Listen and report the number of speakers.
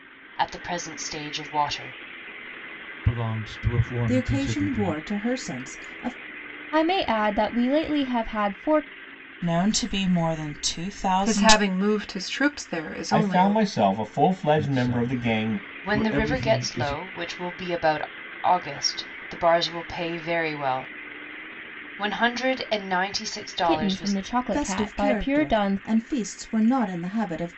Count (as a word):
seven